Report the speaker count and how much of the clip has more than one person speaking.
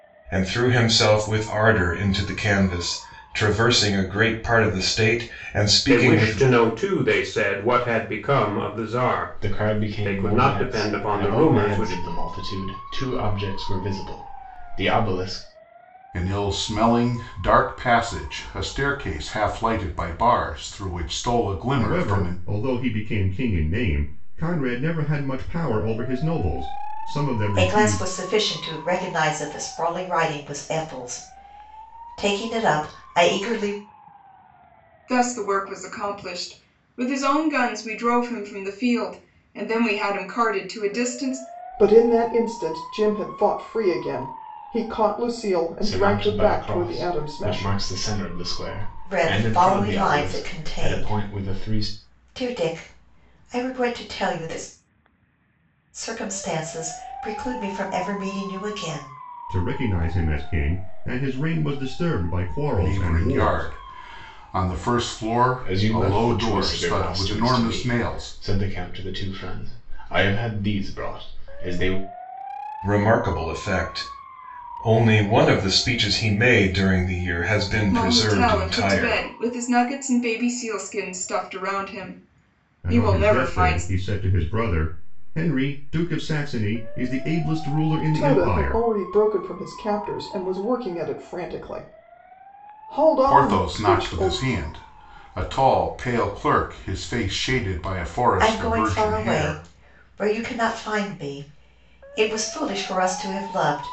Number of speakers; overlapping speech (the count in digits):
8, about 18%